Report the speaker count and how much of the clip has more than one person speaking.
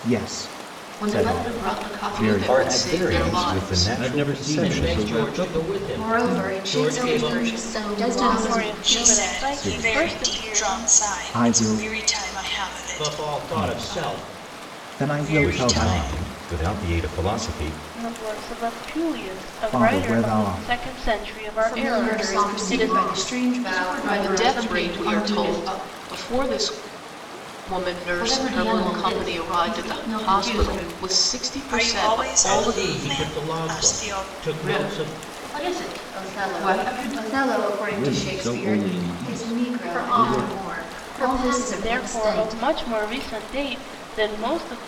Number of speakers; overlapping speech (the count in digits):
10, about 66%